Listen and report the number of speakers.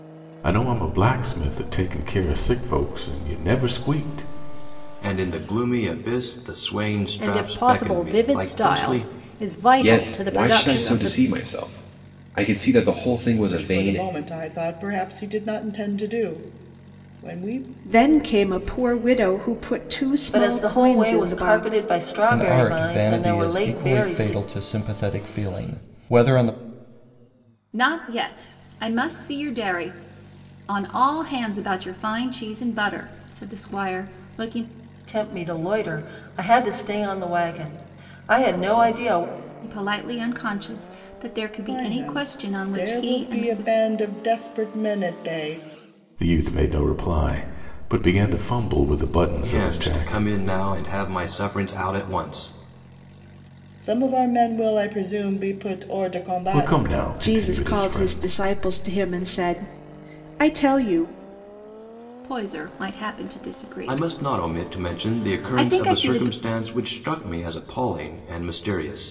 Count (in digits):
9